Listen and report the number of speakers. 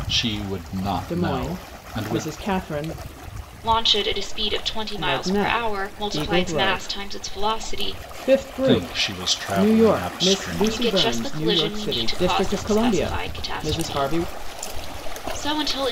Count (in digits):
3